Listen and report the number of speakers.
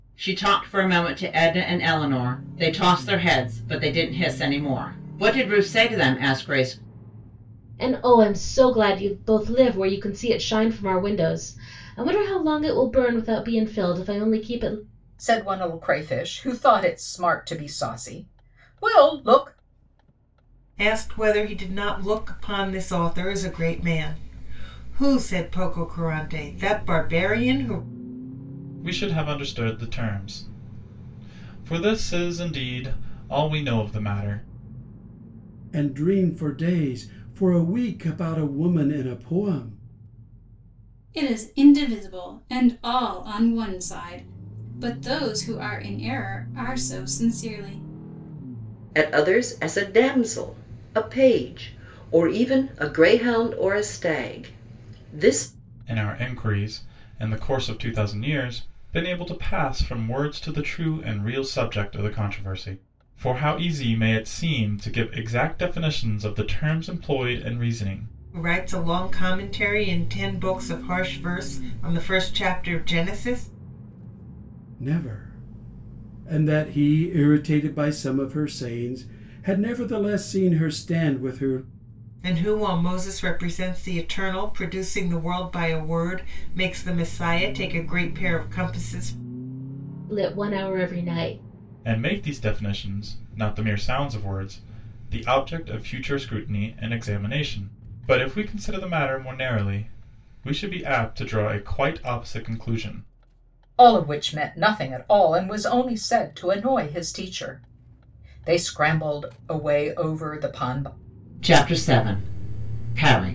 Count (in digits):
8